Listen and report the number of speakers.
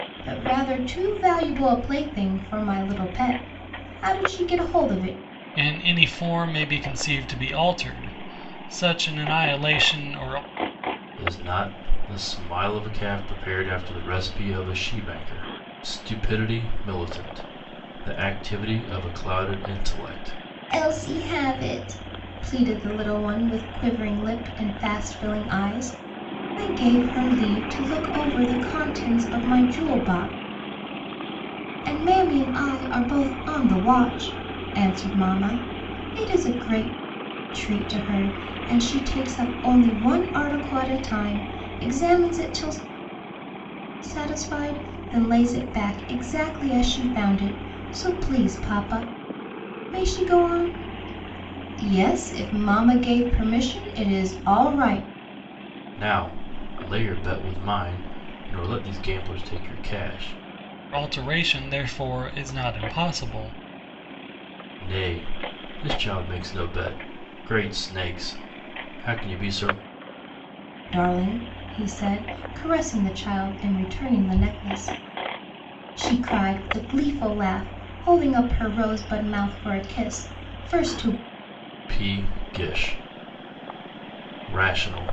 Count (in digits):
3